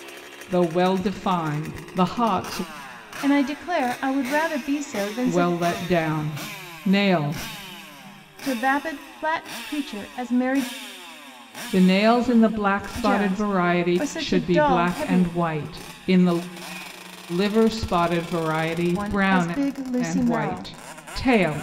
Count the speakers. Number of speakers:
2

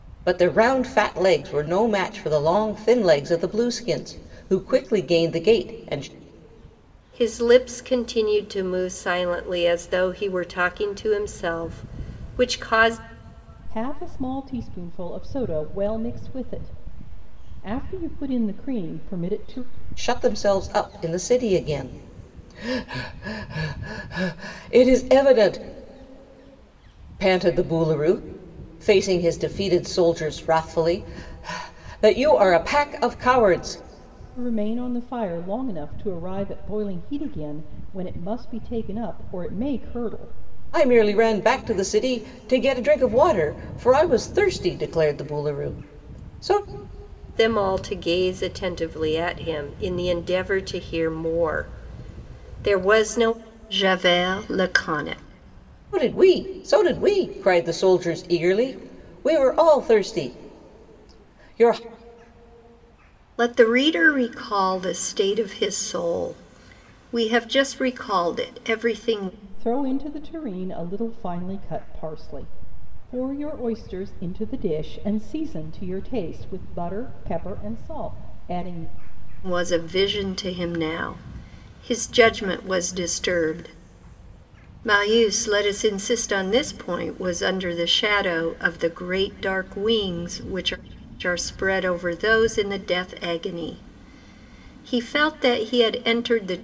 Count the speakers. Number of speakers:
3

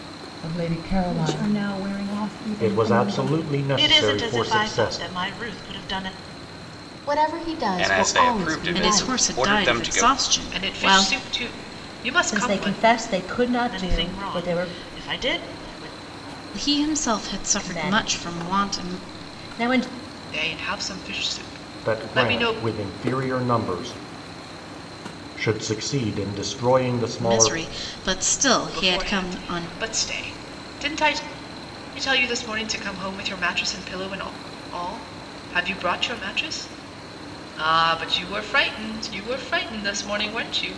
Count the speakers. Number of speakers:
9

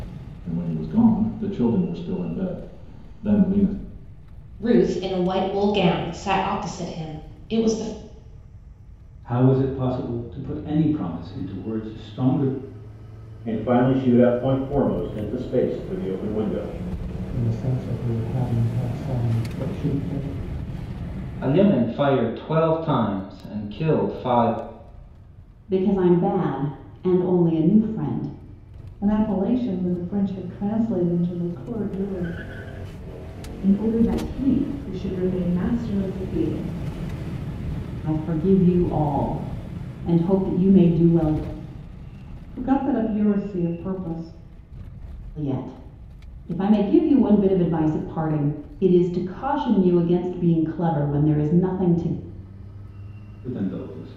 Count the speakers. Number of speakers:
9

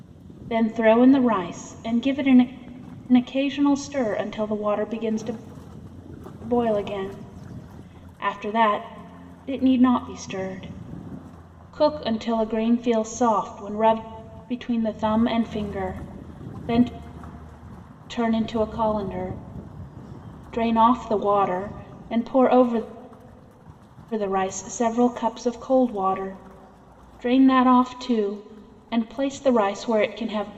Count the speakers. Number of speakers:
1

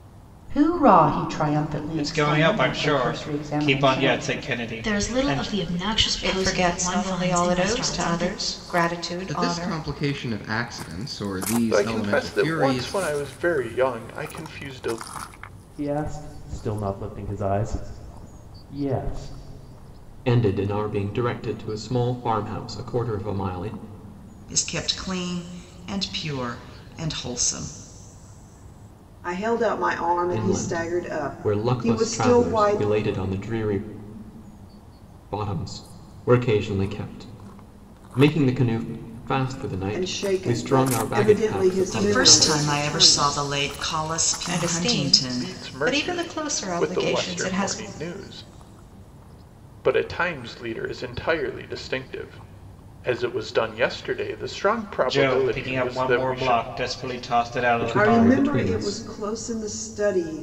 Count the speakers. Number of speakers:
10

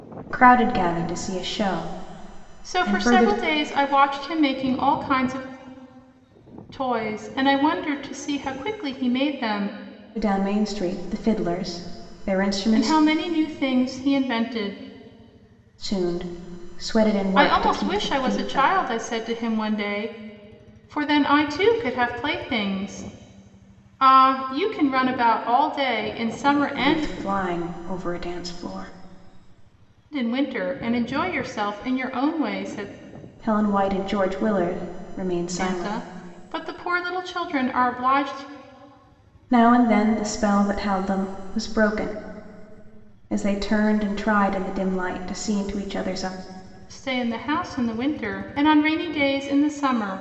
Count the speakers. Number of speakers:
2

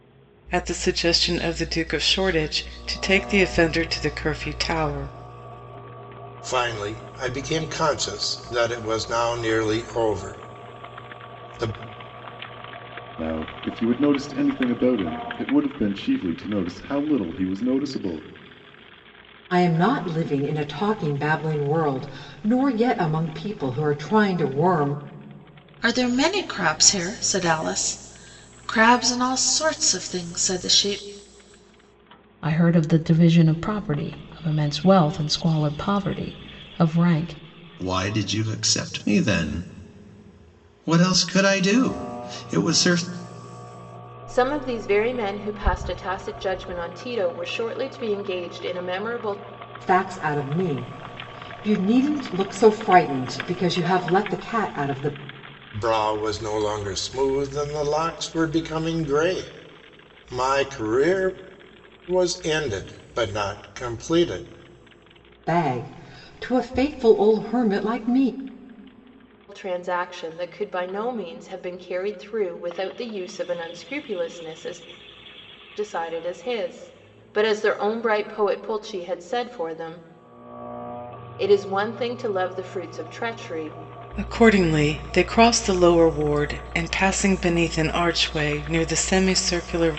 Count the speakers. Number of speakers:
8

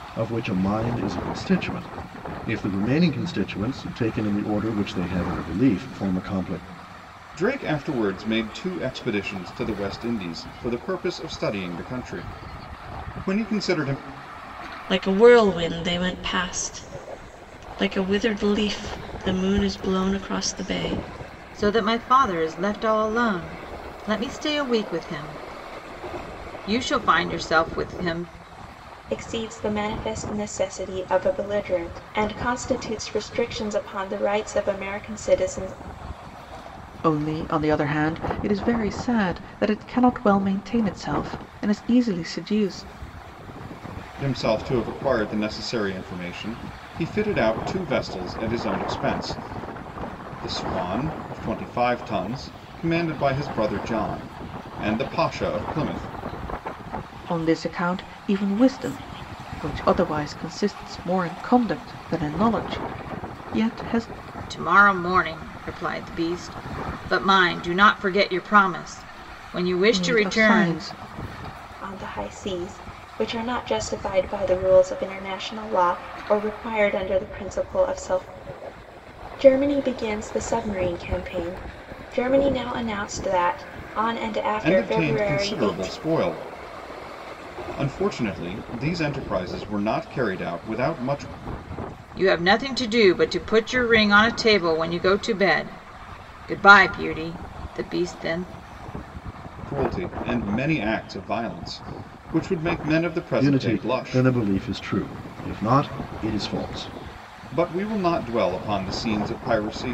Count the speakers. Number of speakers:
6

